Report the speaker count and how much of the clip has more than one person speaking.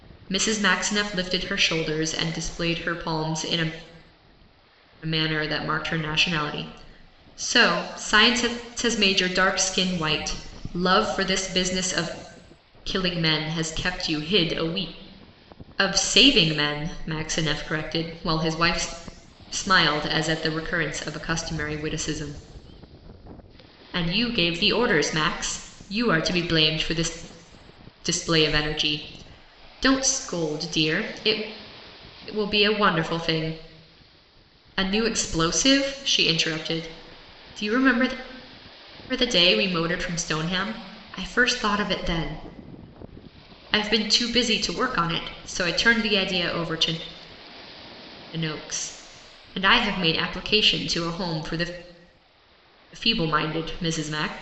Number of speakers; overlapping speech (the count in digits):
1, no overlap